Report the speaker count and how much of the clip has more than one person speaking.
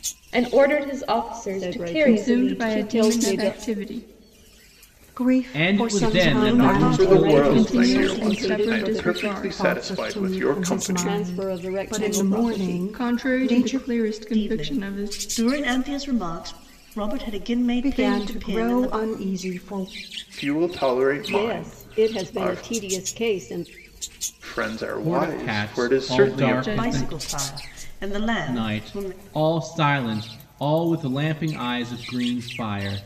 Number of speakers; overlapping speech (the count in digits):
7, about 50%